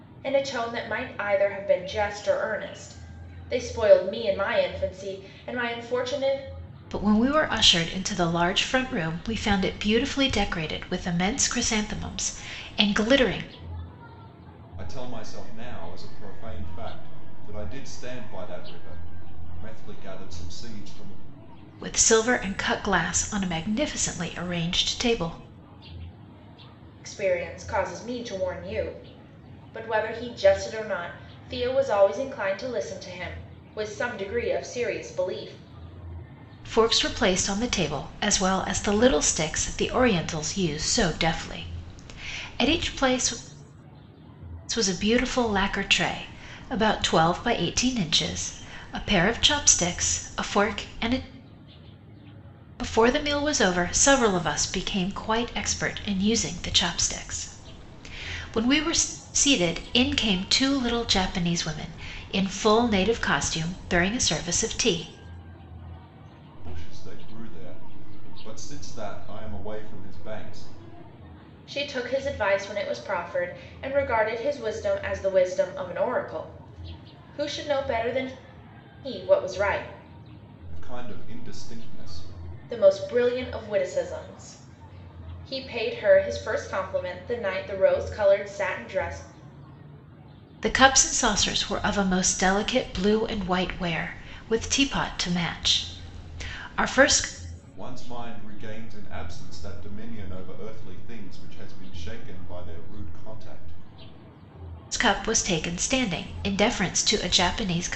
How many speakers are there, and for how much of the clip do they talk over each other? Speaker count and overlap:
3, no overlap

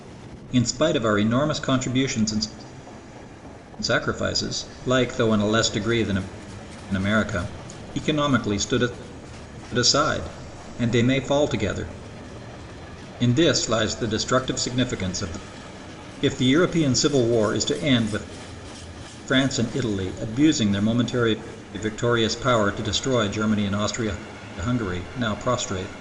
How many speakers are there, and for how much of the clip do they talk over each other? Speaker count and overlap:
1, no overlap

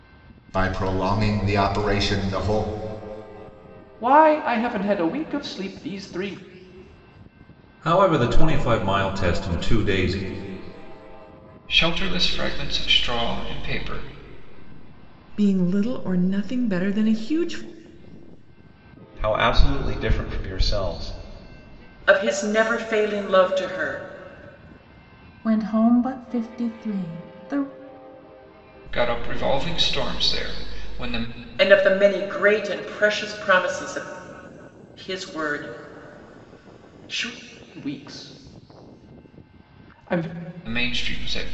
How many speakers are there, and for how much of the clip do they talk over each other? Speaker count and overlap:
8, no overlap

